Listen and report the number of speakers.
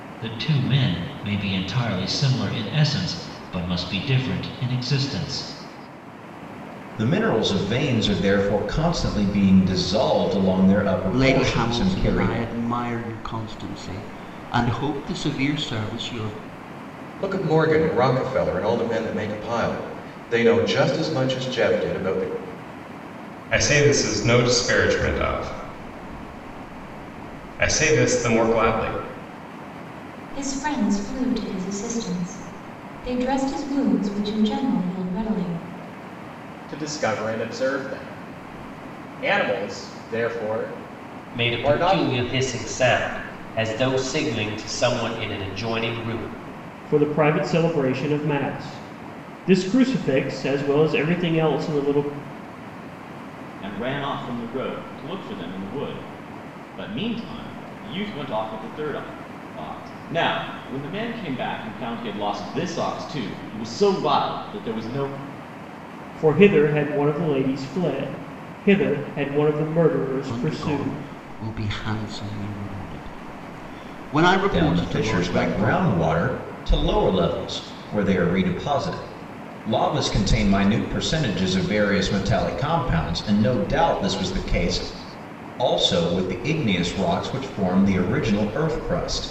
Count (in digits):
10